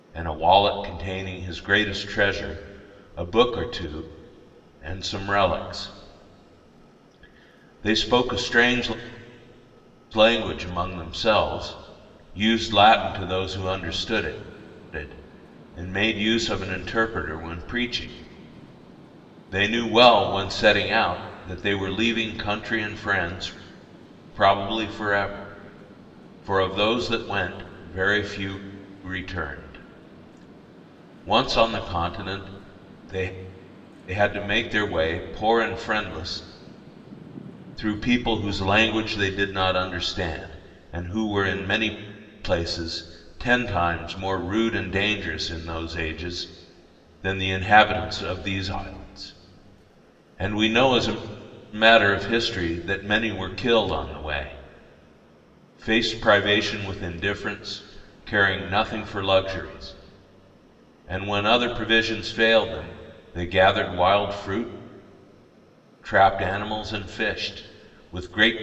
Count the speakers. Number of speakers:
1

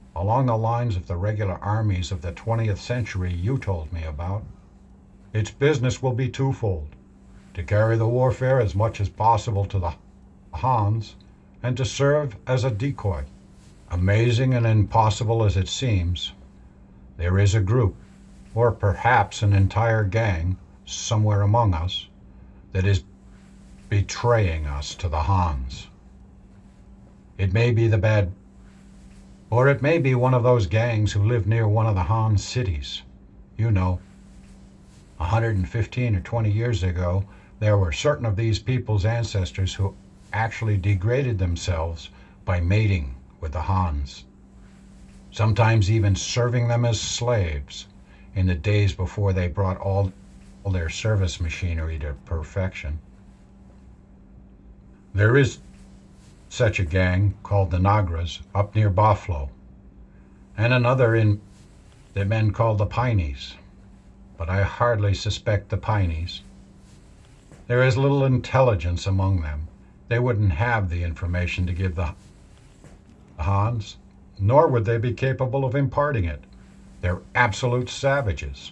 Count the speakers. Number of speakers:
1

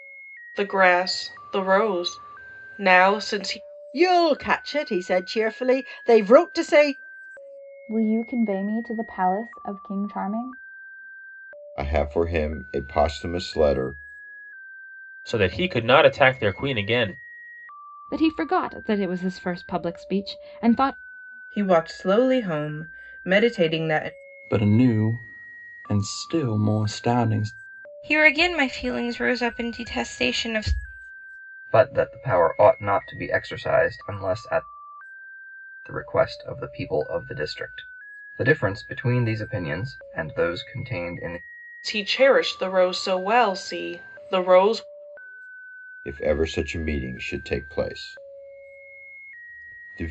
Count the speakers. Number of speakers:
10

